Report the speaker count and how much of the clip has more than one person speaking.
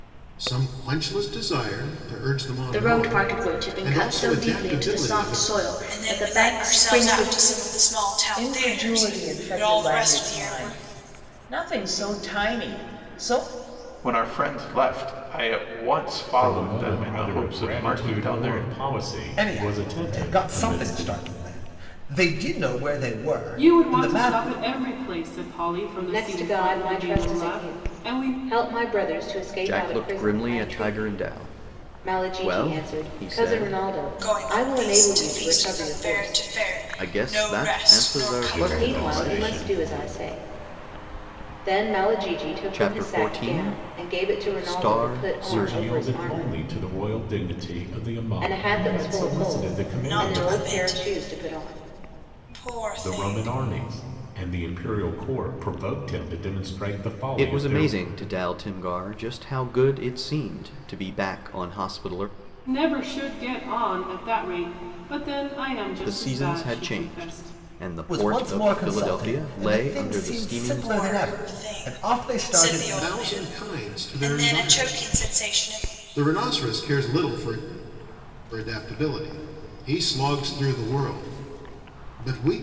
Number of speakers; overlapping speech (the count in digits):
10, about 49%